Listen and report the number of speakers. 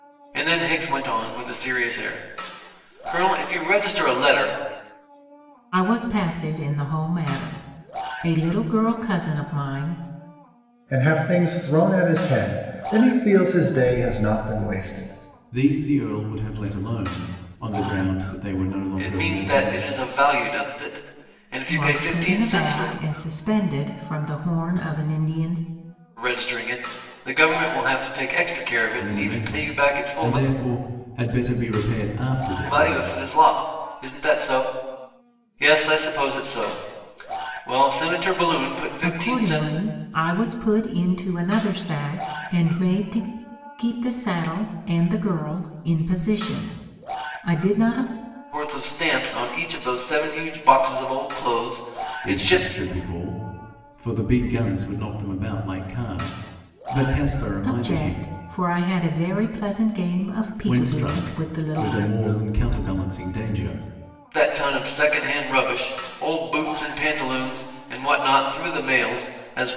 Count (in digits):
4